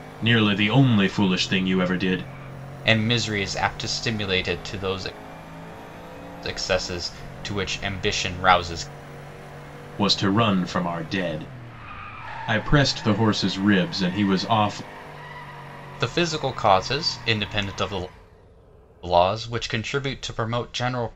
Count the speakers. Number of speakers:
2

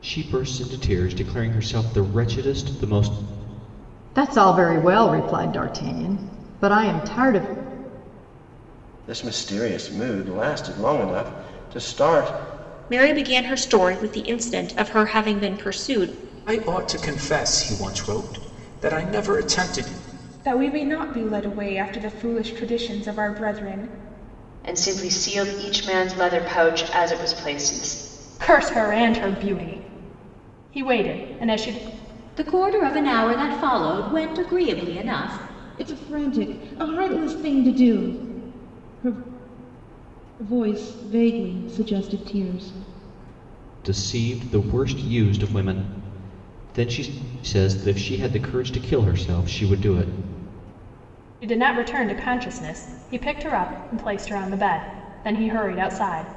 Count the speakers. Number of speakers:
10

